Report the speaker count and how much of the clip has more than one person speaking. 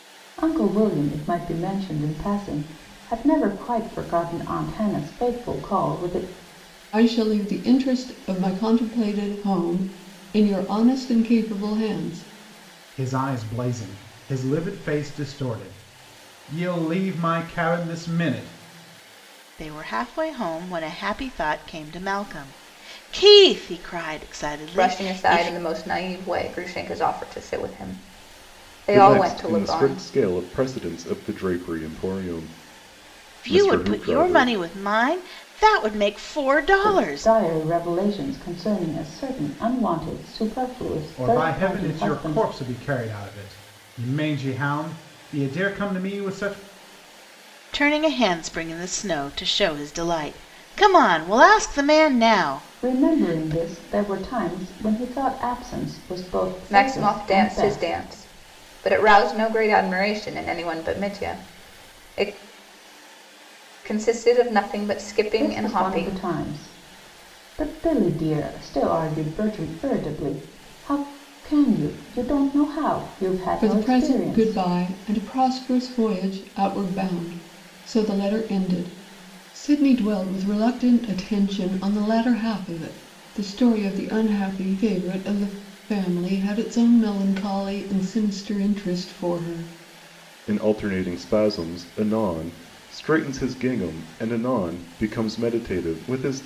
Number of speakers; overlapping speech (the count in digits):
6, about 10%